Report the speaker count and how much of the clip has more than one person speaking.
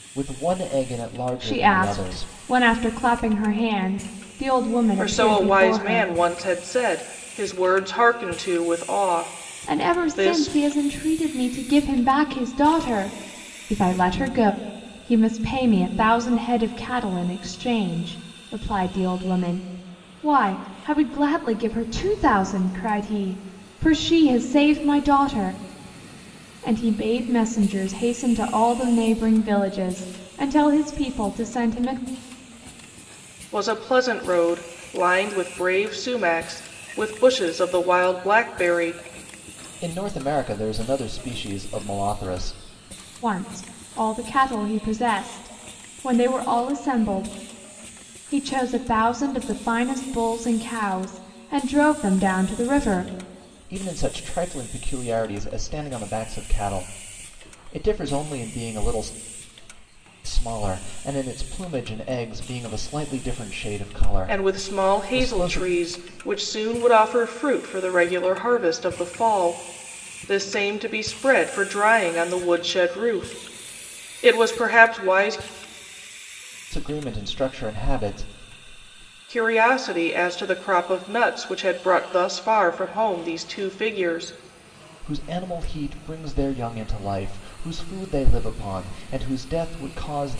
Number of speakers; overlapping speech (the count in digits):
3, about 5%